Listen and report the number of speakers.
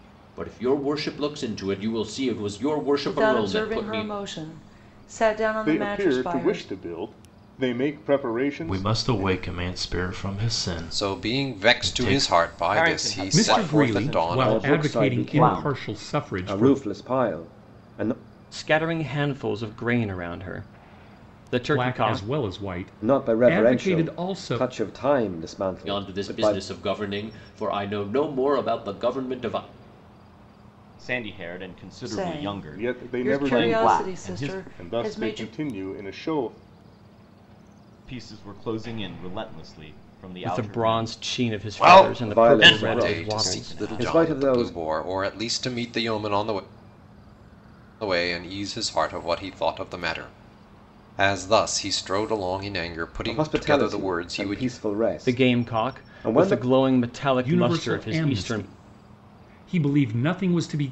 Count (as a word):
nine